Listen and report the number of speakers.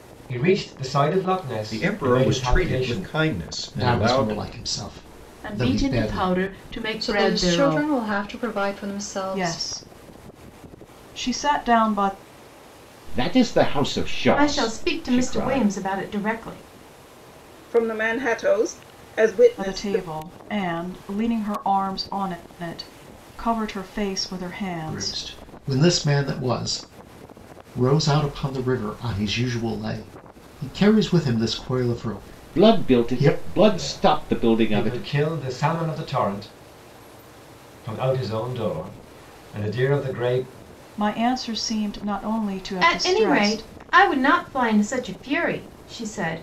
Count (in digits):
9